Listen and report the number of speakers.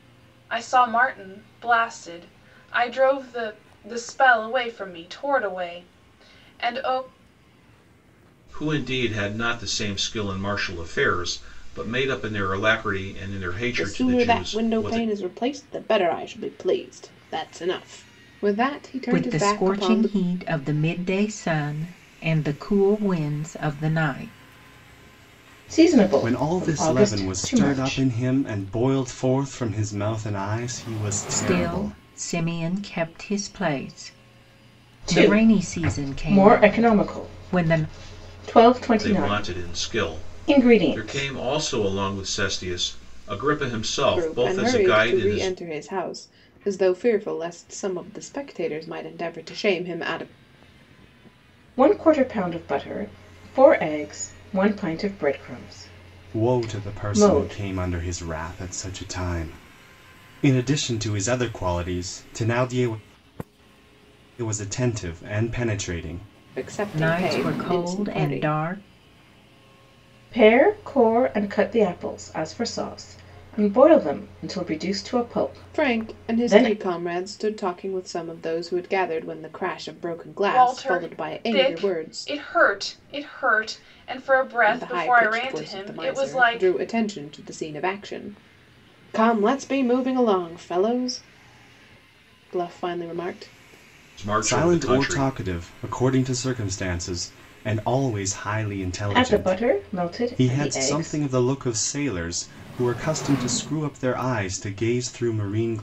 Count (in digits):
6